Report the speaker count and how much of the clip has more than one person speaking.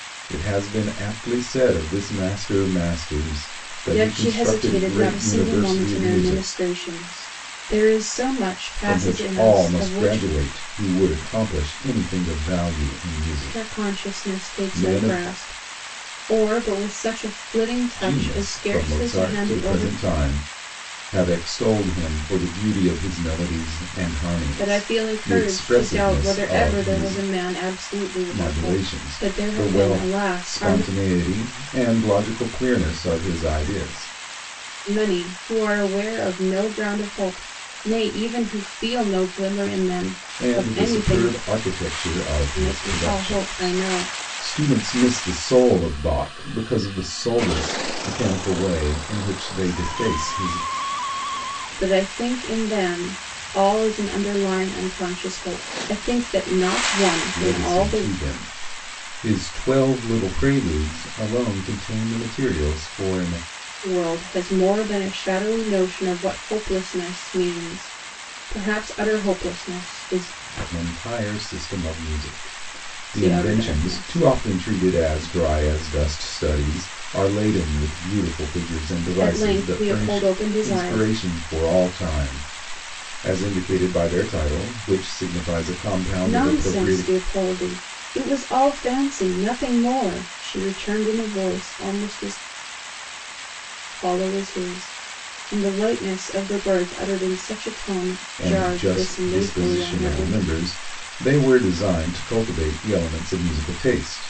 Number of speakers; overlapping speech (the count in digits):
2, about 21%